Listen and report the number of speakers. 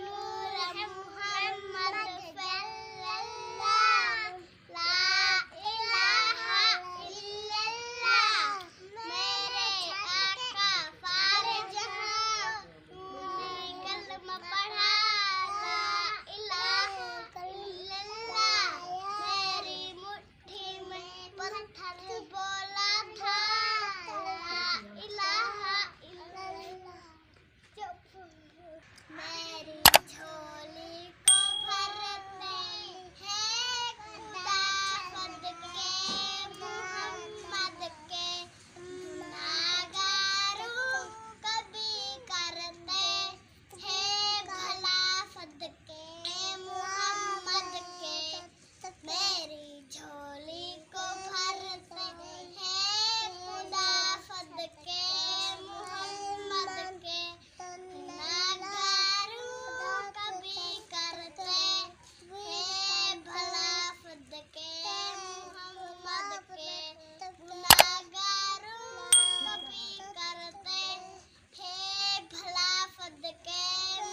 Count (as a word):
zero